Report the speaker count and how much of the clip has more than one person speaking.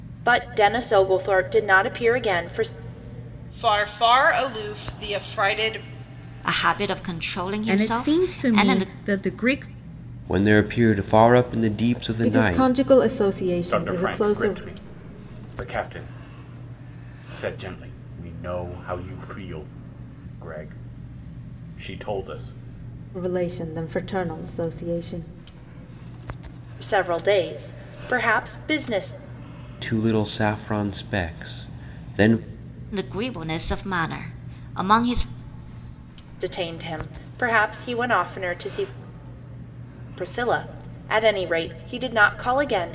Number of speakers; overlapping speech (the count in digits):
7, about 7%